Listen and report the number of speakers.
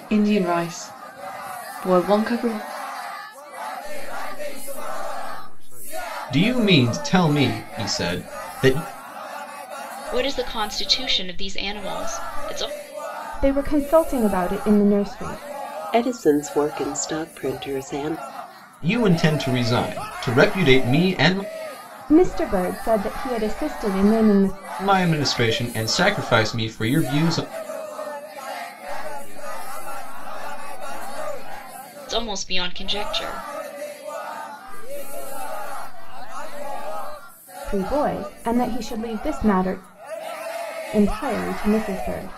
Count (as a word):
six